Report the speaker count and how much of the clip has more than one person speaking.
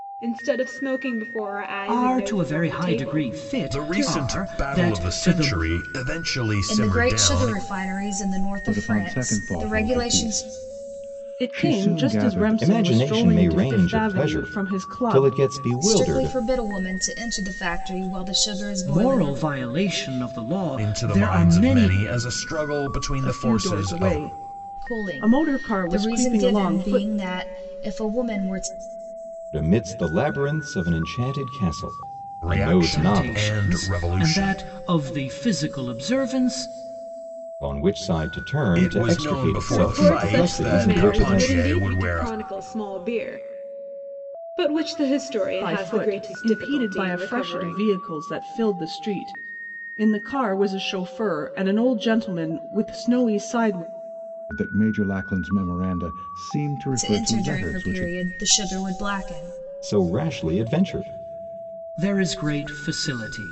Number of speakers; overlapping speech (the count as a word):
seven, about 40%